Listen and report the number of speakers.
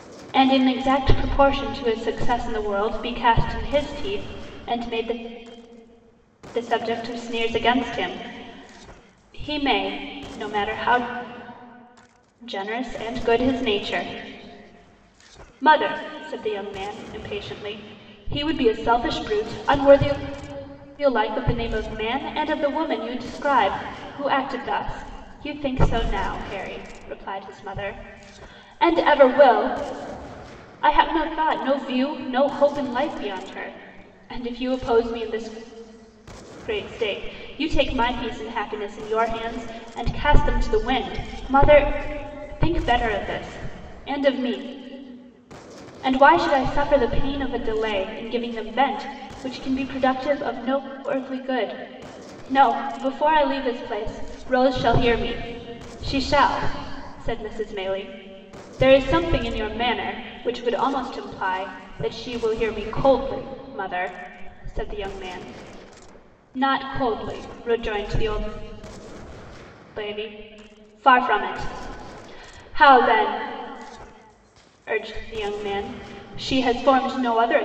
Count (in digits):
1